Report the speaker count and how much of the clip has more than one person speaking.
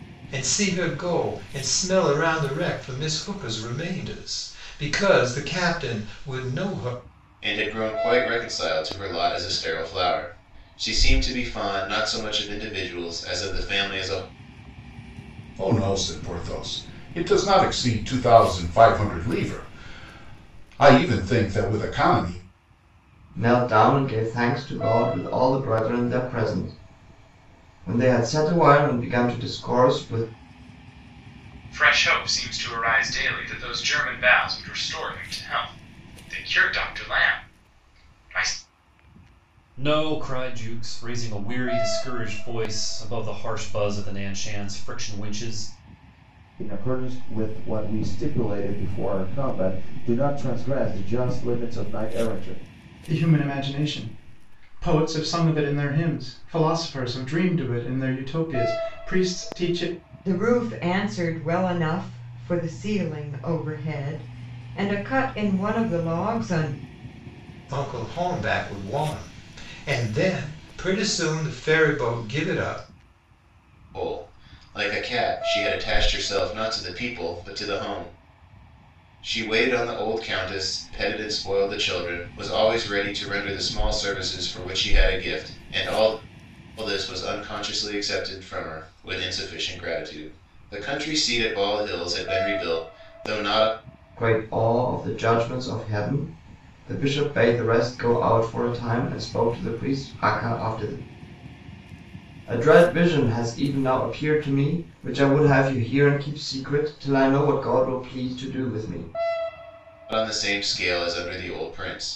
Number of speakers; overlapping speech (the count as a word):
nine, no overlap